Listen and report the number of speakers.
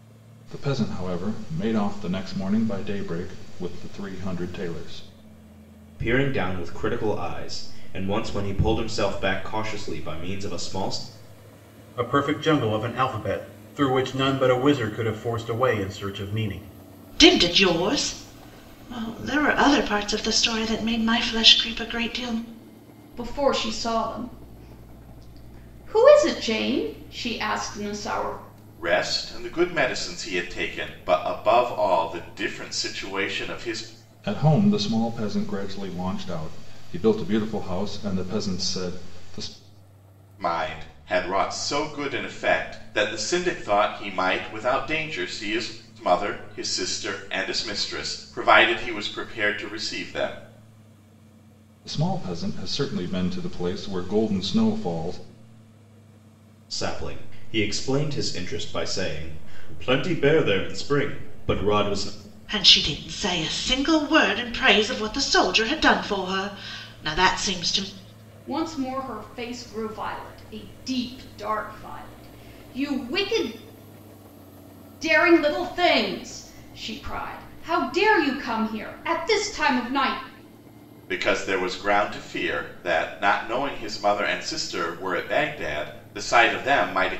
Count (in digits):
6